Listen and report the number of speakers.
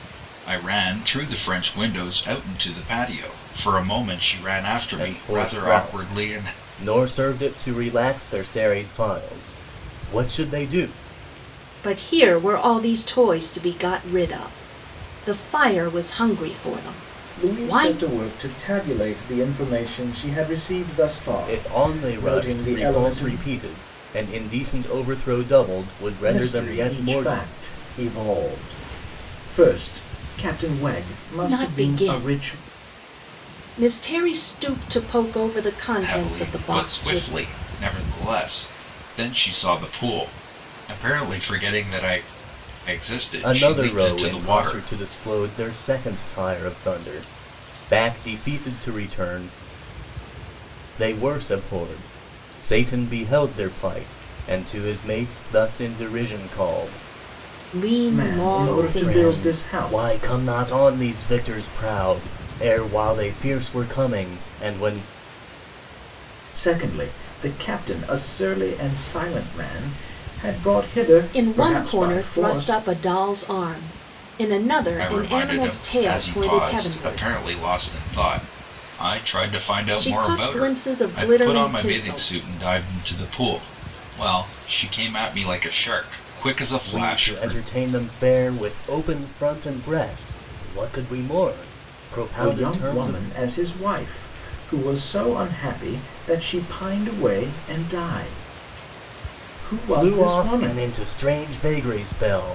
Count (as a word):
four